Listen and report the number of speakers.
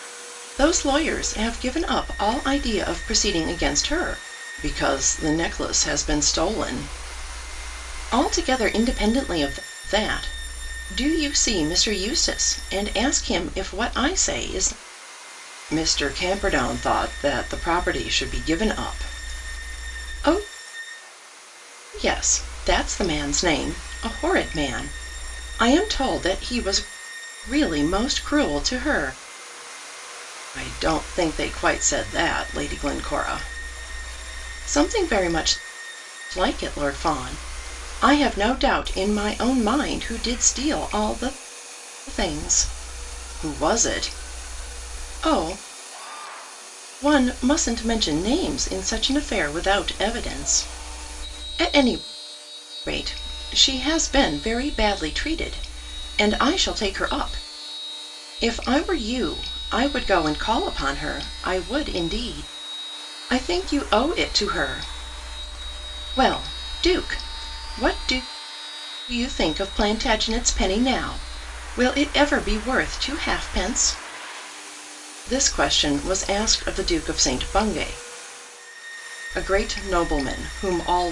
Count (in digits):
1